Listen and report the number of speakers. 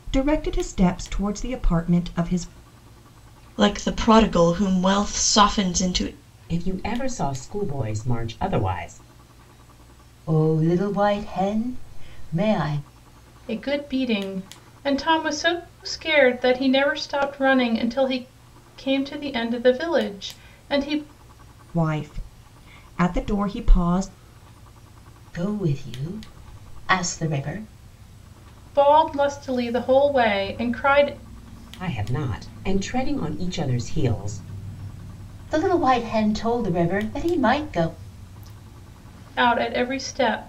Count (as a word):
five